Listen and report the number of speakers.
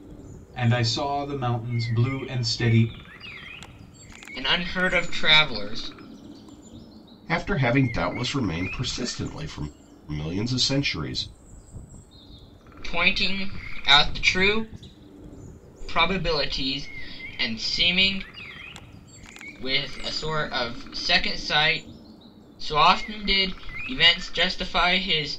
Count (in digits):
3